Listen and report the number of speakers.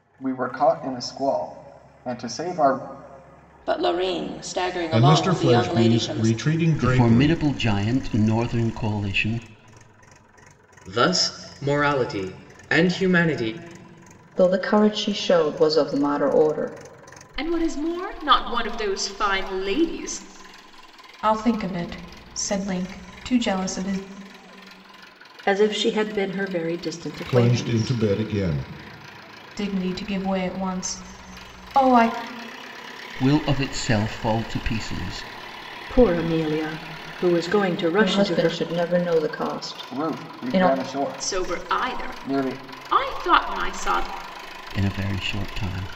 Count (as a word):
nine